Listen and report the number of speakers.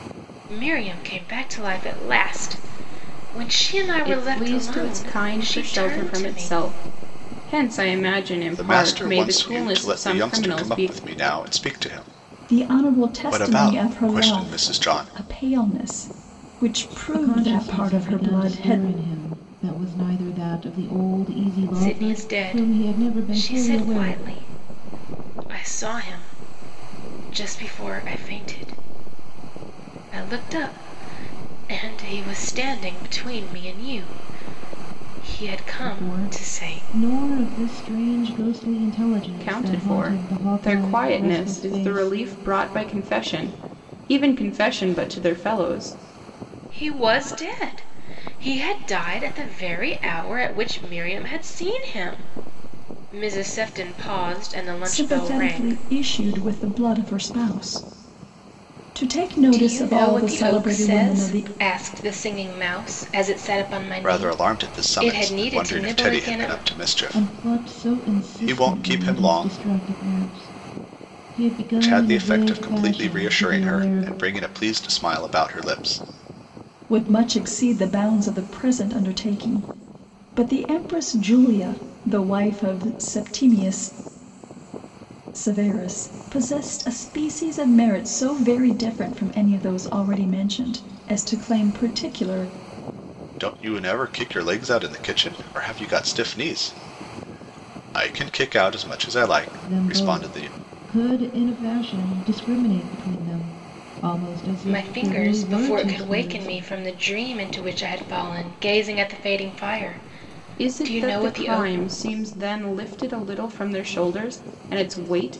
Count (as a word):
five